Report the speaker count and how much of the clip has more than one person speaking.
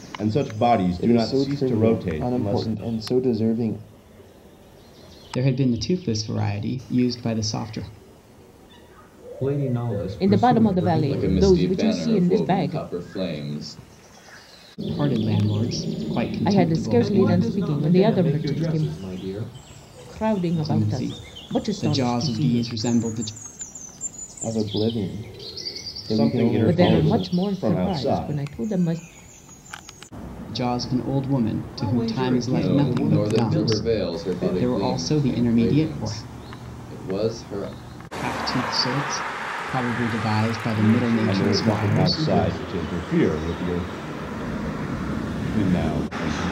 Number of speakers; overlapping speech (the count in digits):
6, about 39%